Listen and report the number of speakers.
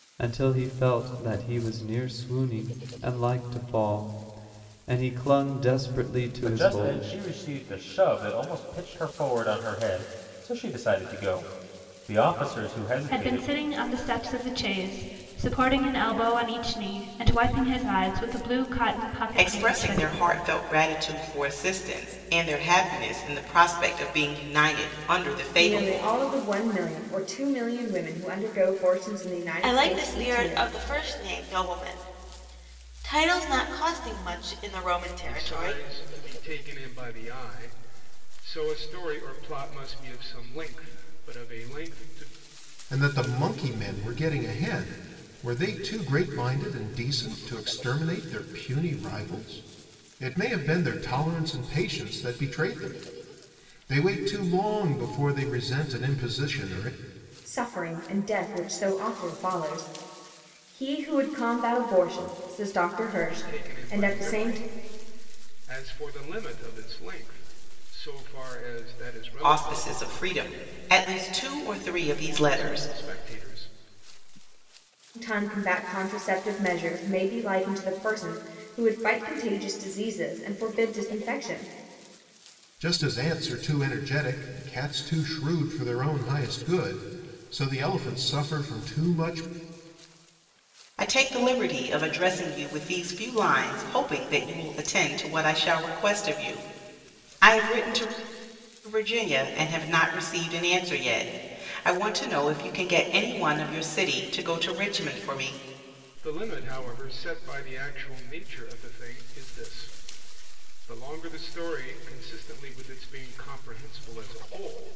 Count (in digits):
8